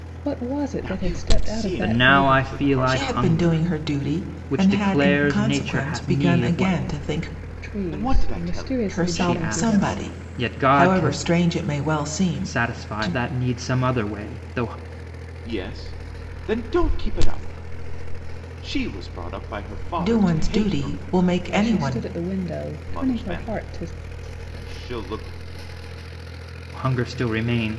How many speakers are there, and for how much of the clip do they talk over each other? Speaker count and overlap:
four, about 44%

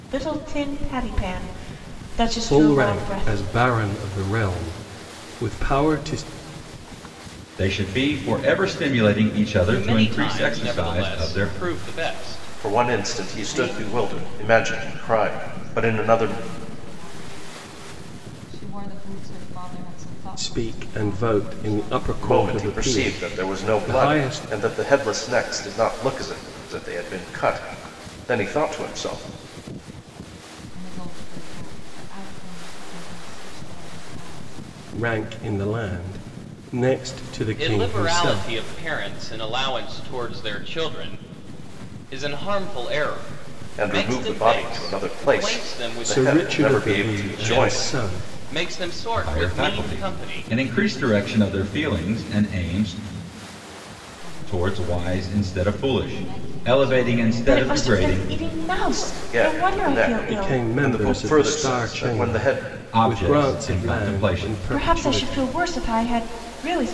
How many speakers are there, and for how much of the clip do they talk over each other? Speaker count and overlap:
six, about 42%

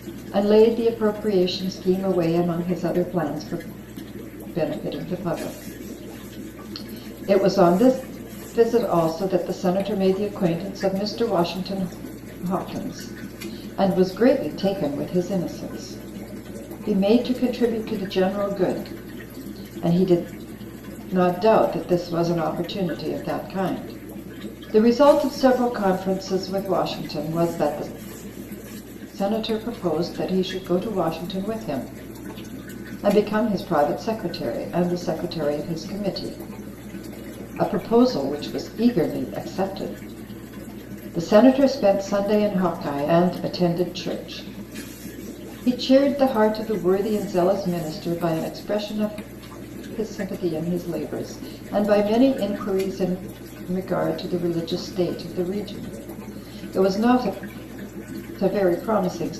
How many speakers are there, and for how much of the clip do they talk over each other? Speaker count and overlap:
one, no overlap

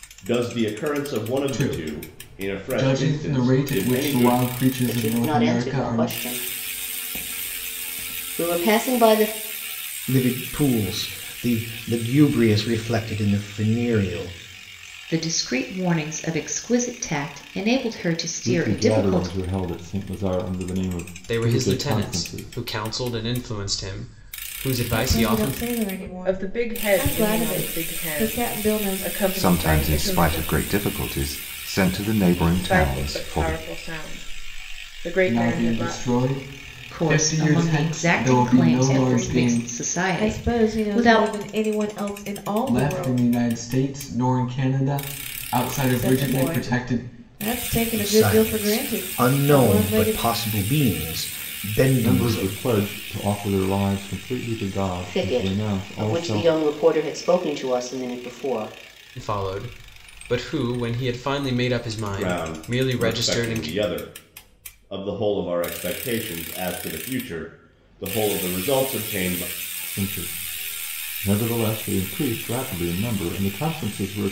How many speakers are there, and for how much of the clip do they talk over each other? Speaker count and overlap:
ten, about 35%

